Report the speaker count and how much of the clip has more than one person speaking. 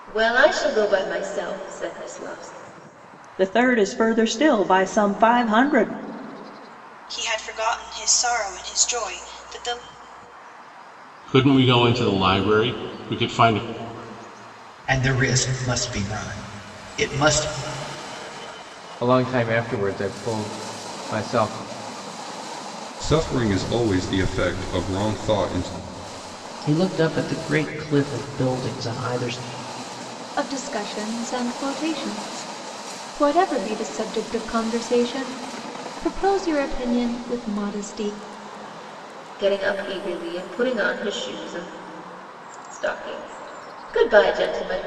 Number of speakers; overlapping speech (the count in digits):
9, no overlap